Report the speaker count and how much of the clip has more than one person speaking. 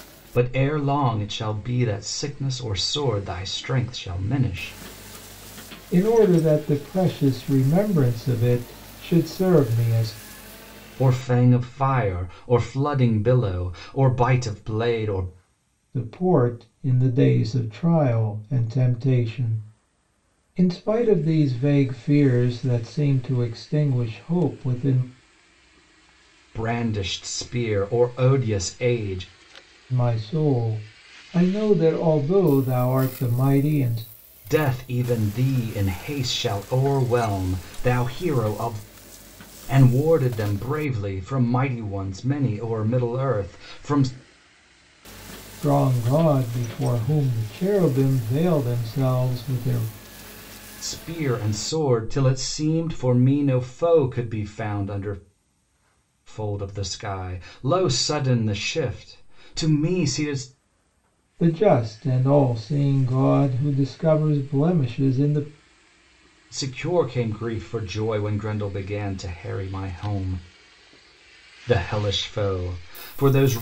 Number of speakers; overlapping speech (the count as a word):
two, no overlap